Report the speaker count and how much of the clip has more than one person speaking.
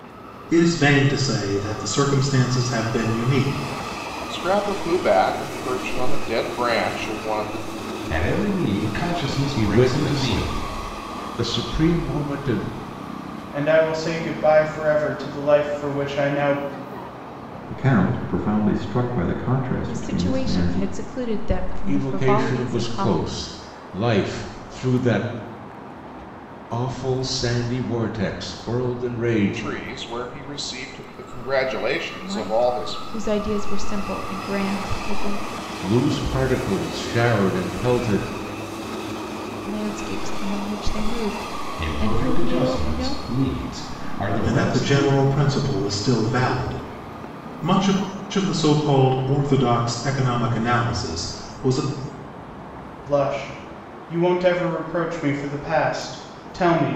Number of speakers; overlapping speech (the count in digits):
7, about 12%